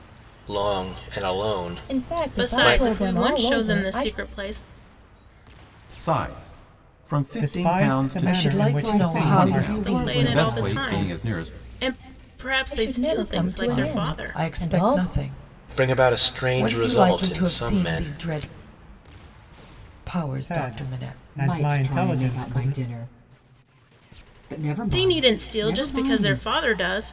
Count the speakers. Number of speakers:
7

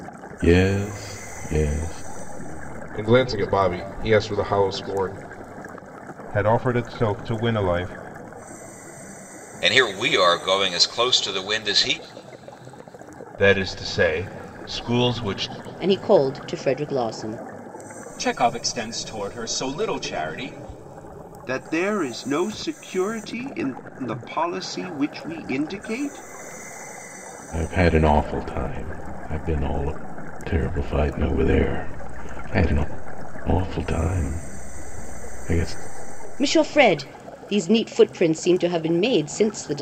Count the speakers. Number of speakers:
8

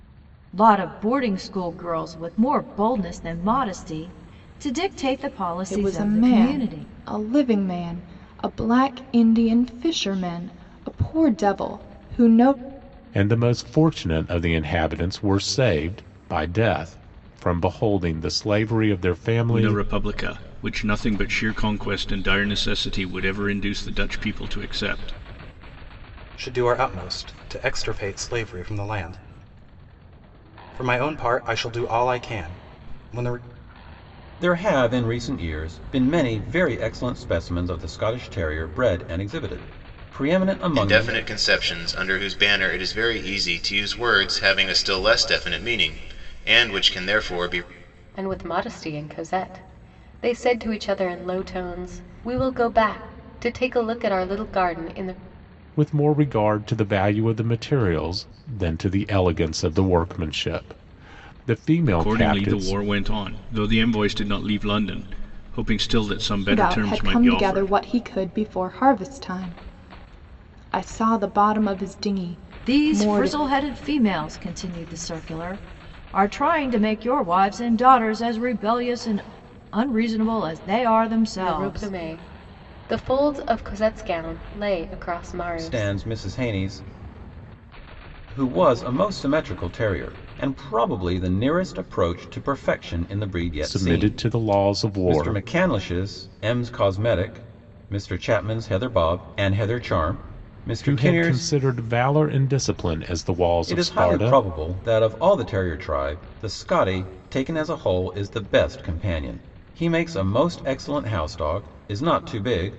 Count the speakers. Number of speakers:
8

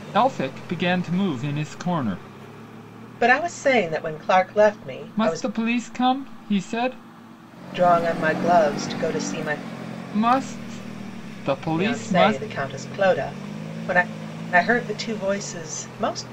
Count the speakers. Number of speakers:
2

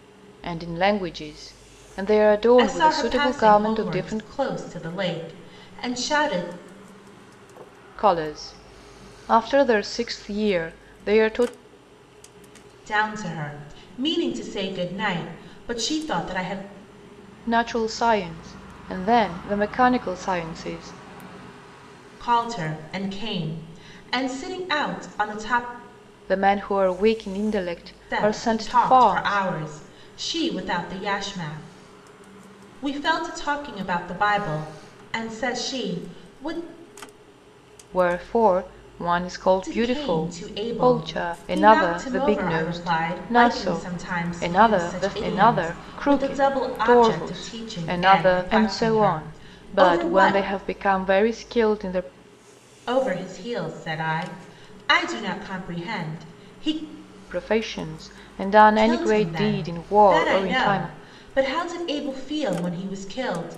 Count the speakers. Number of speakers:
2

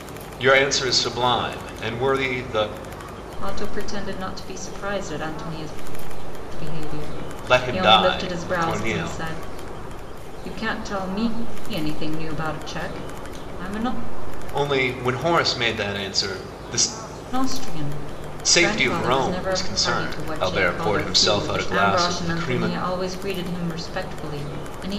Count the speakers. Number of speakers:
2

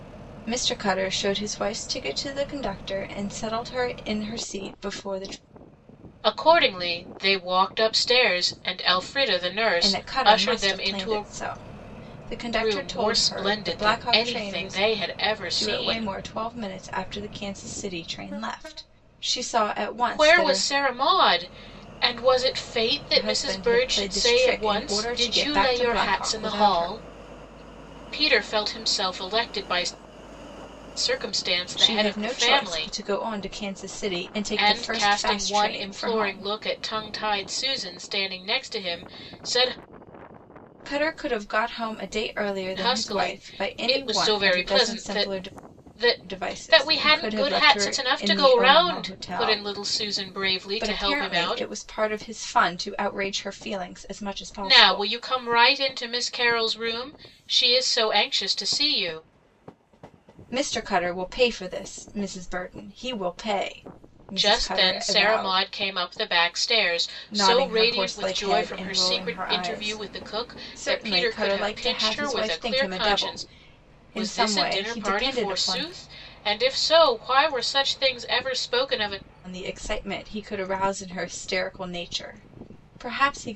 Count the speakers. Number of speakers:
2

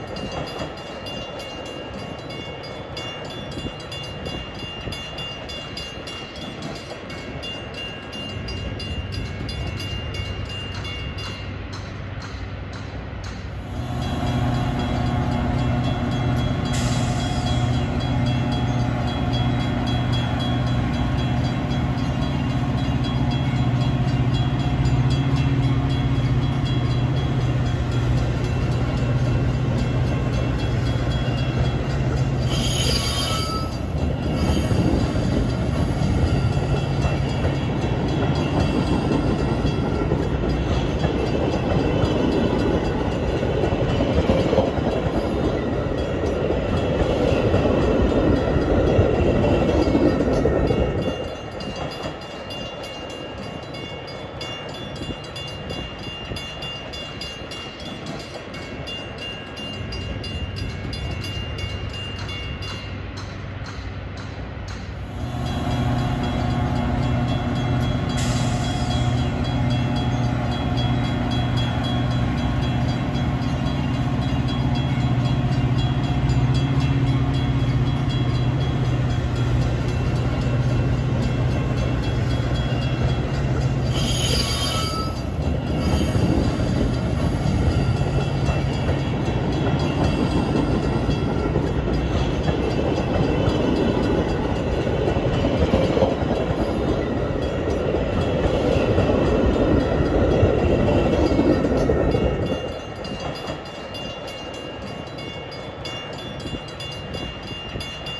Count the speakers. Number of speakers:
0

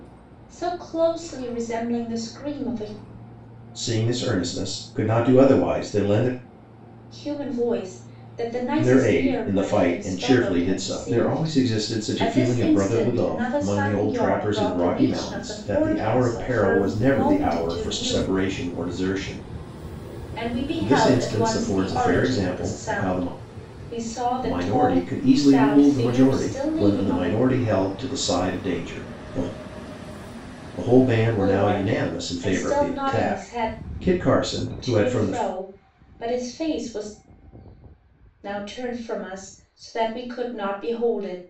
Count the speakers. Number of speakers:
2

